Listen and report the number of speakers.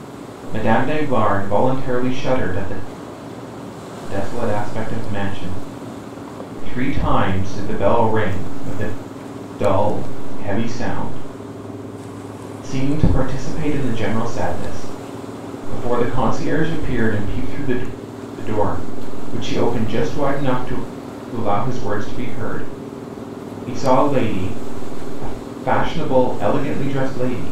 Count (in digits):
1